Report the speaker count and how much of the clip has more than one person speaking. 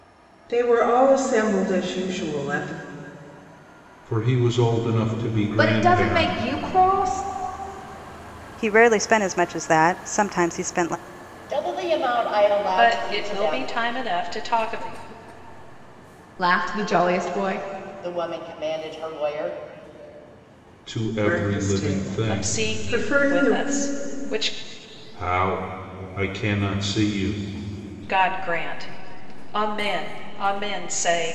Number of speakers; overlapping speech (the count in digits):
6, about 14%